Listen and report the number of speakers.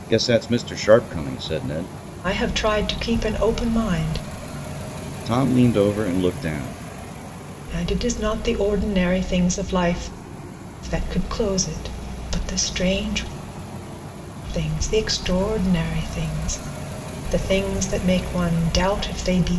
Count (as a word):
two